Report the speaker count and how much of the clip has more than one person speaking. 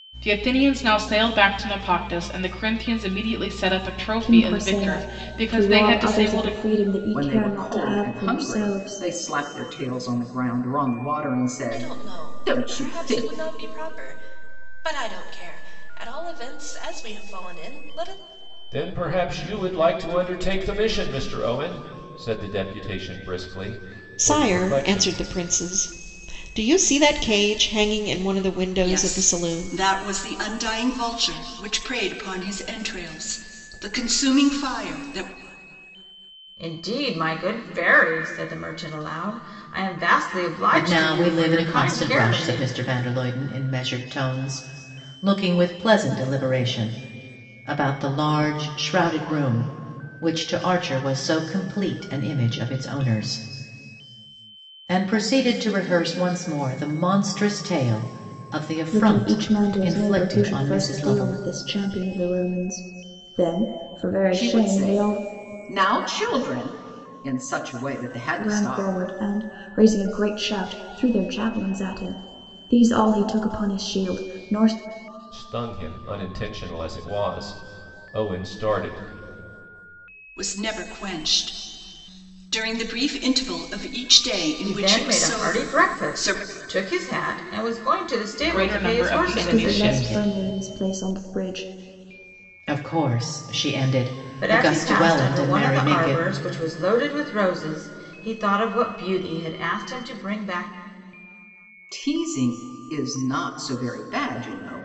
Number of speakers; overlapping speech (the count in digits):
9, about 20%